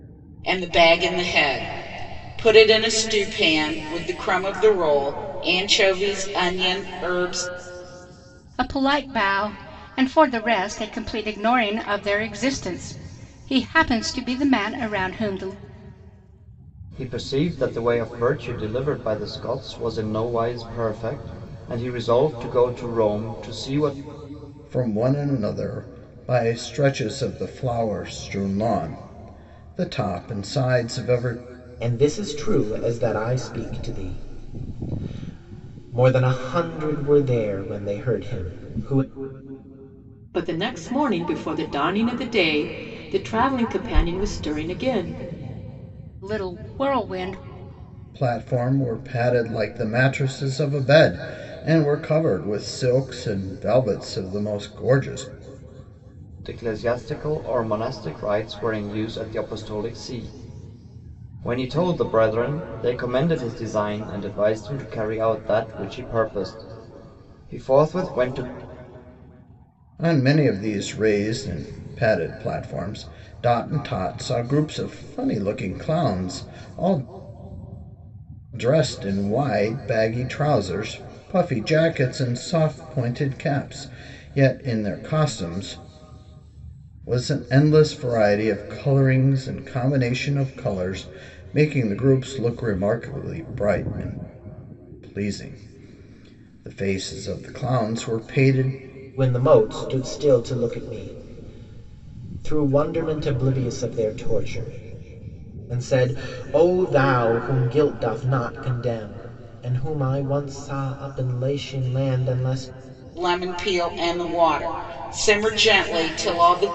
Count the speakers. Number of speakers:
6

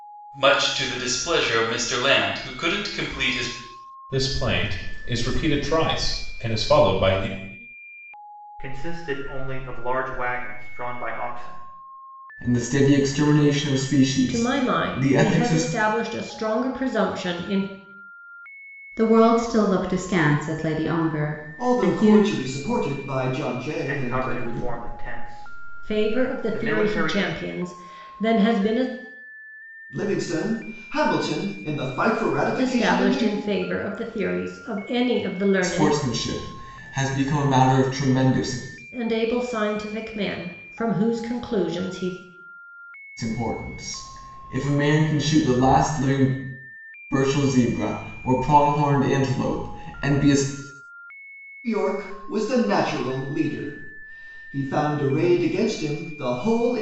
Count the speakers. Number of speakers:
7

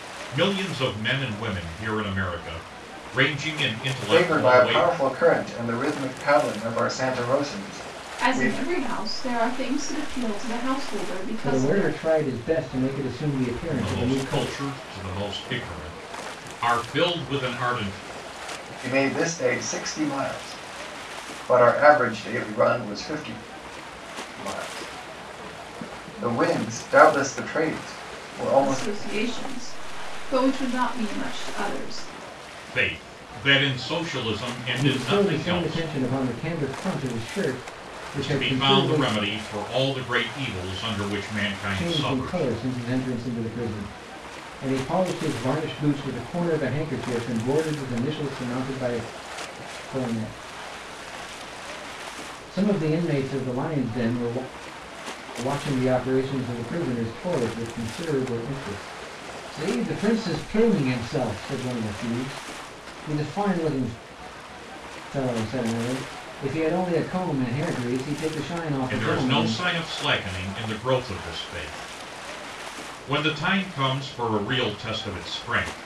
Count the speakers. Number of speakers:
4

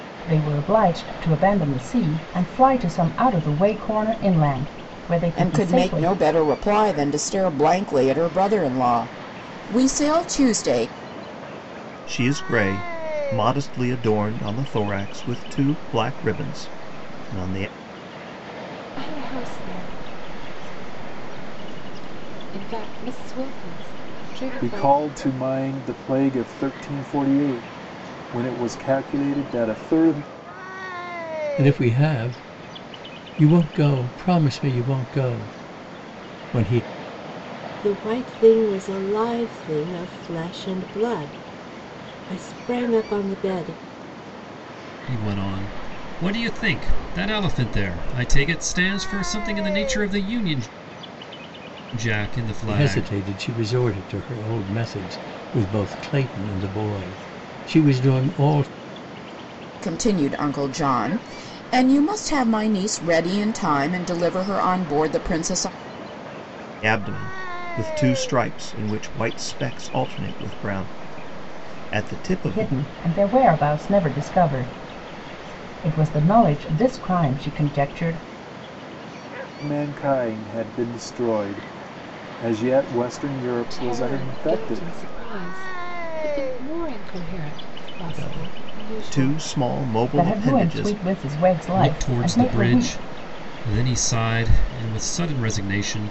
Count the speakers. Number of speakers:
8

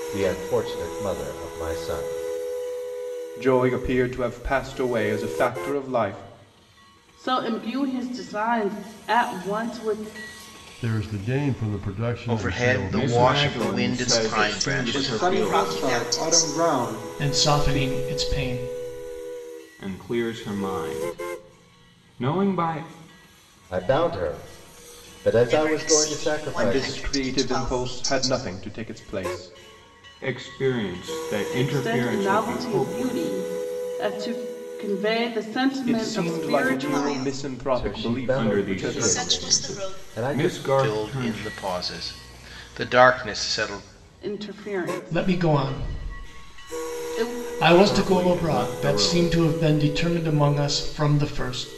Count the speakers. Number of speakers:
9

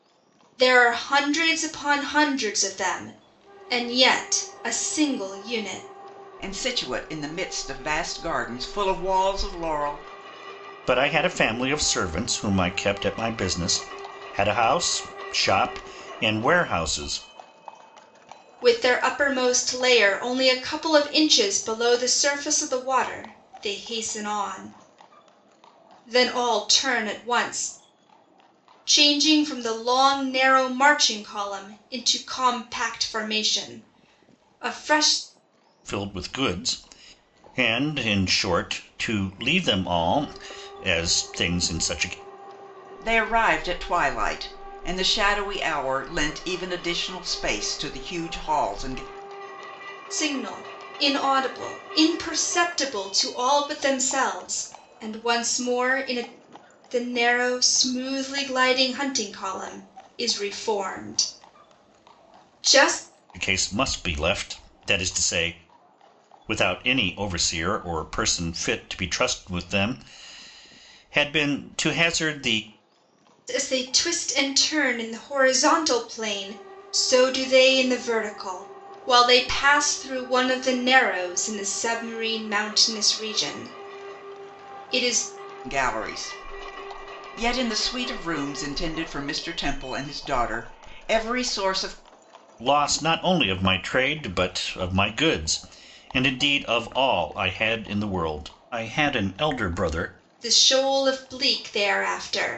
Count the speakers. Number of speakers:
3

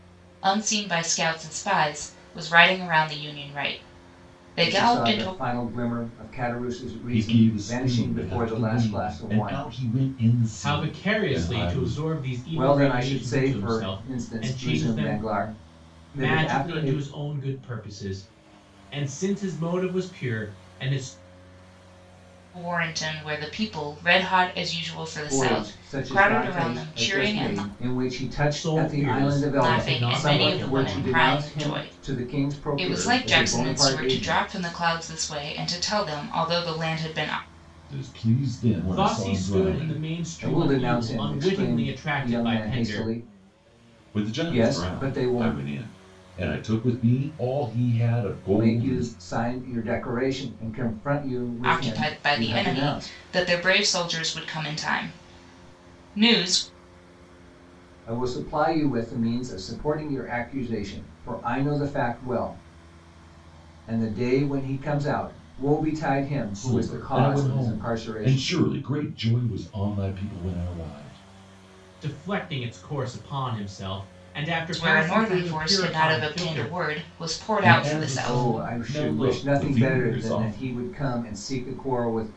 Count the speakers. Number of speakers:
4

